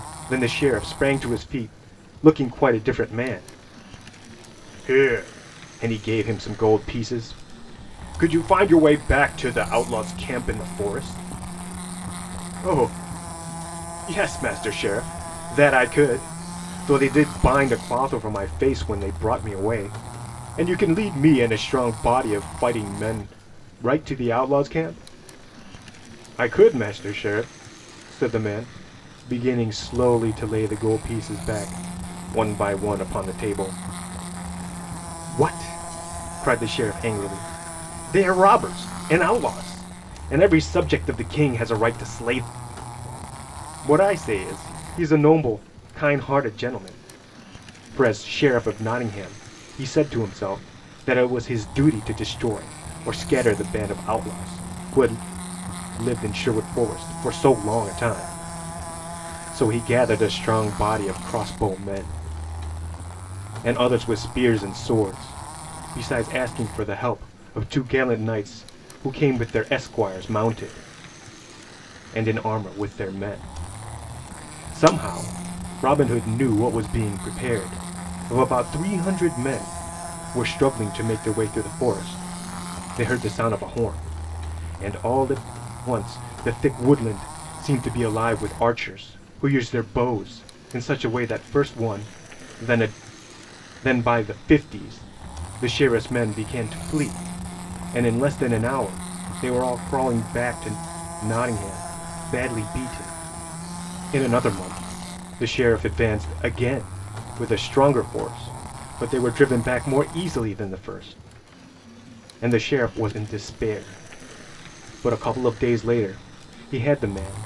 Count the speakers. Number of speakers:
one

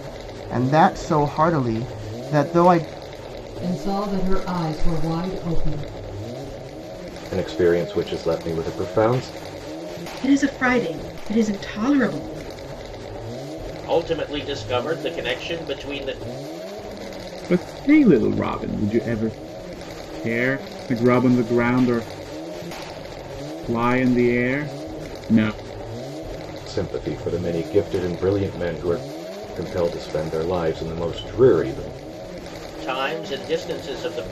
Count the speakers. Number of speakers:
six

